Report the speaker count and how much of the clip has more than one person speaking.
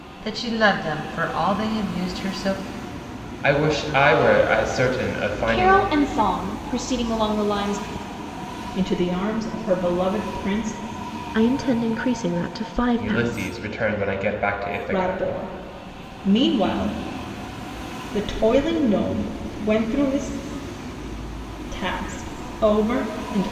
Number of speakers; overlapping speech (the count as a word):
five, about 6%